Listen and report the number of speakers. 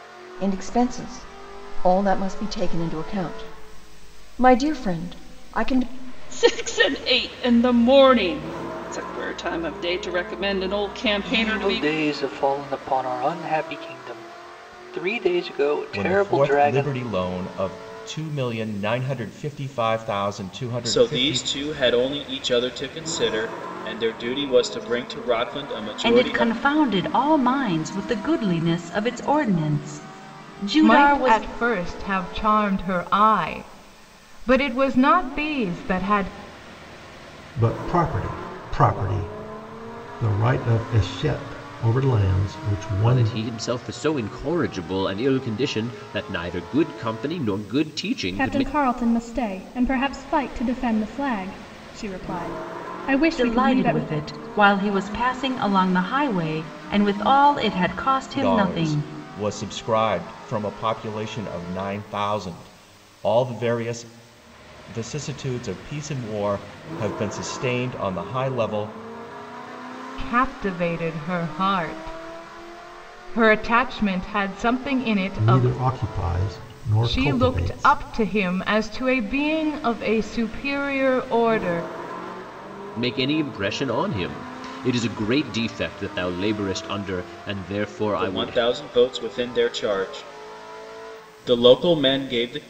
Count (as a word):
ten